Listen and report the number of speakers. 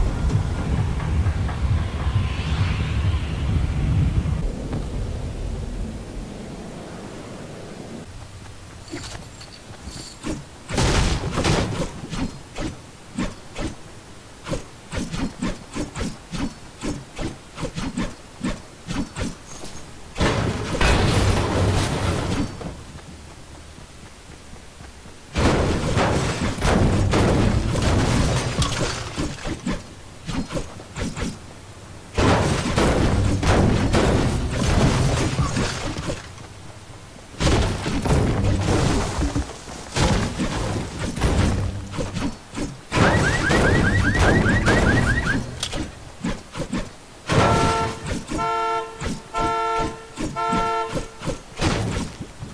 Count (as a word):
zero